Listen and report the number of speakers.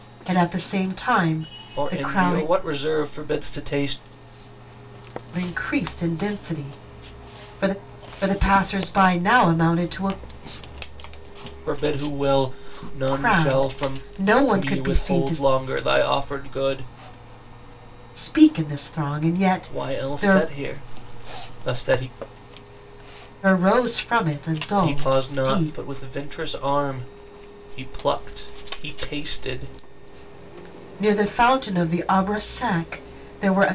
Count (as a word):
two